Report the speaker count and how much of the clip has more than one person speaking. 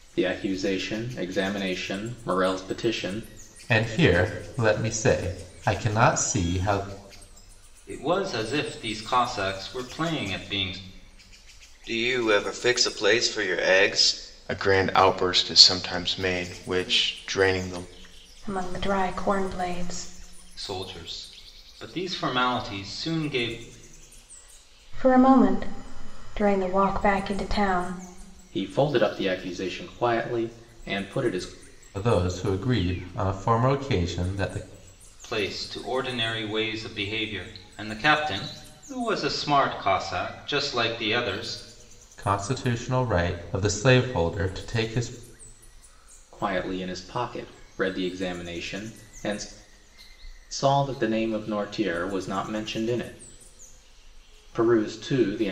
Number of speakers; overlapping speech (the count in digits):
6, no overlap